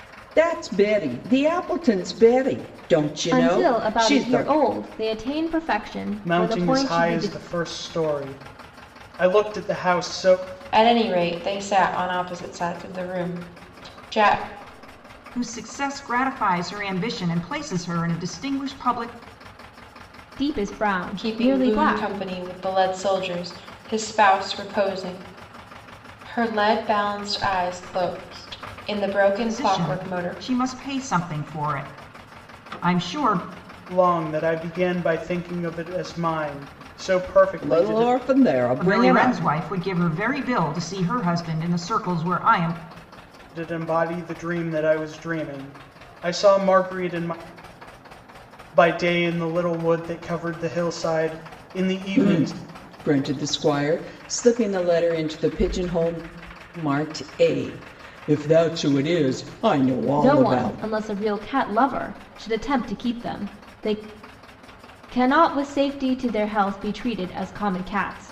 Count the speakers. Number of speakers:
5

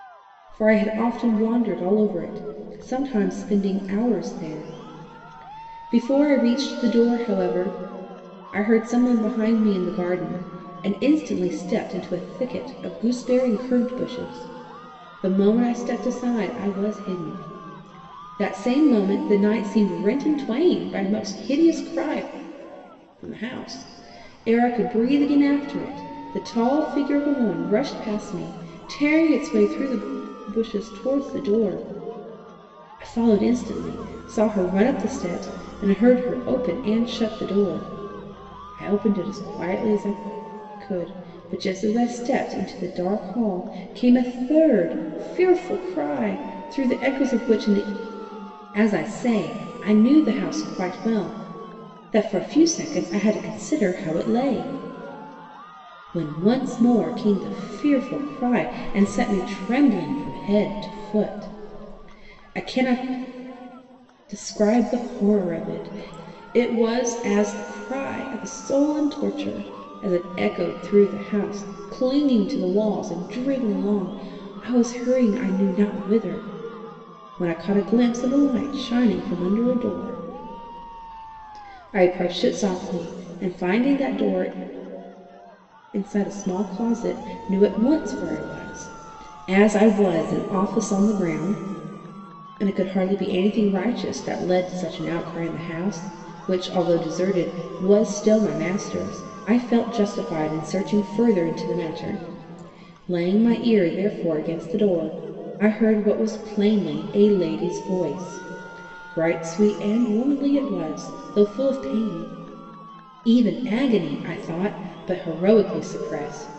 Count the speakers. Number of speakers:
1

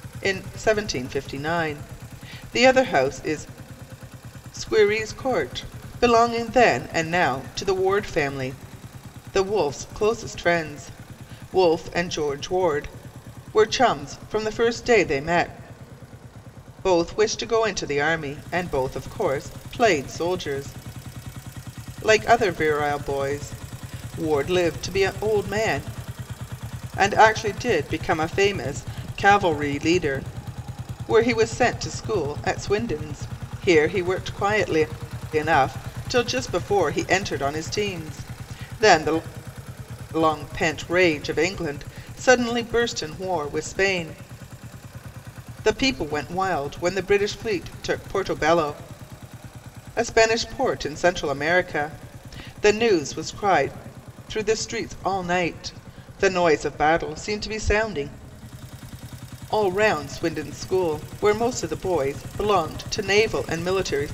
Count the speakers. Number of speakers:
1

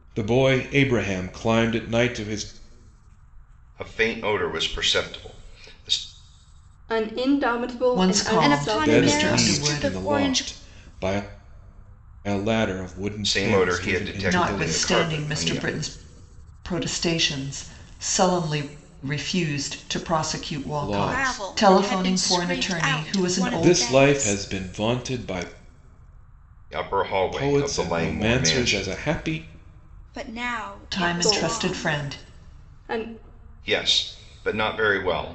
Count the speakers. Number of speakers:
5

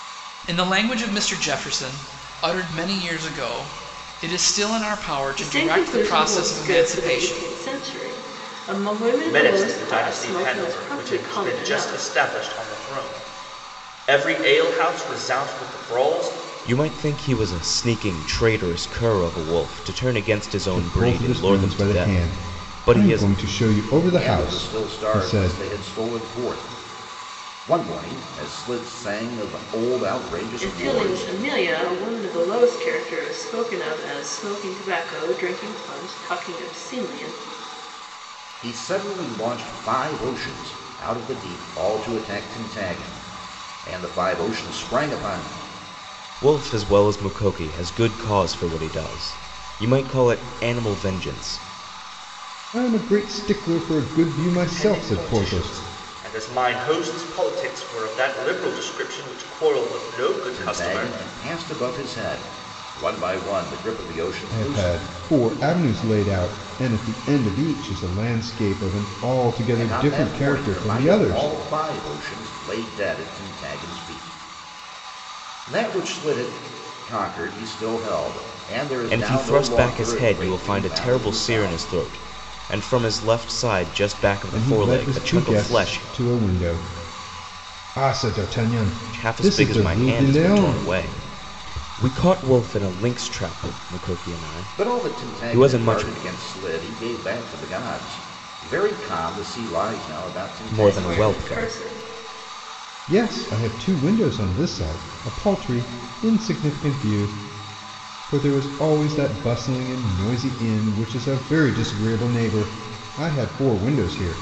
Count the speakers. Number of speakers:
6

